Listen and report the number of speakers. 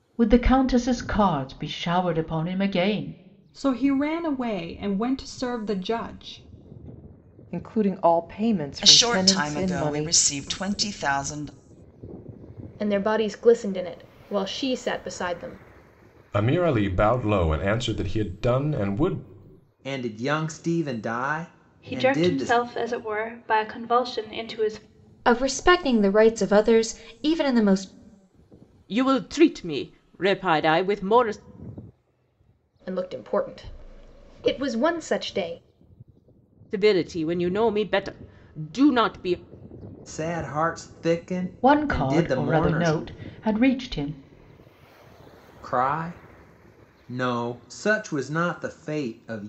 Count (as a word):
ten